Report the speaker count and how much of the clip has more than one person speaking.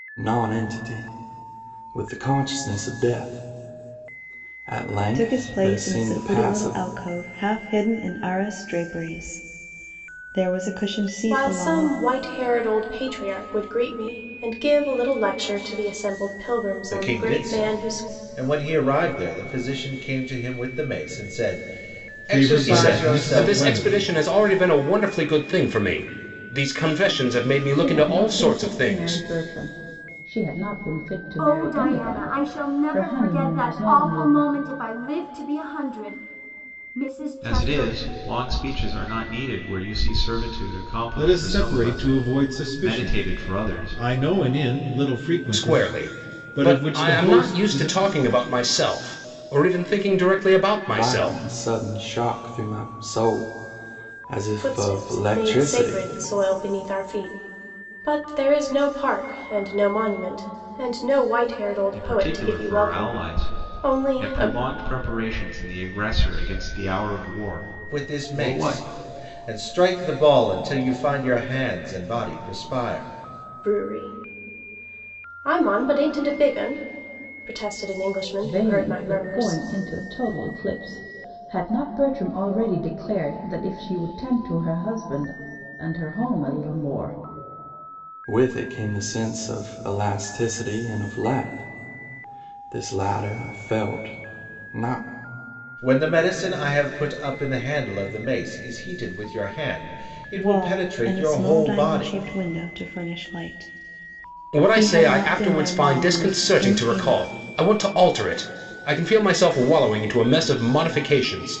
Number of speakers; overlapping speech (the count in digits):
9, about 24%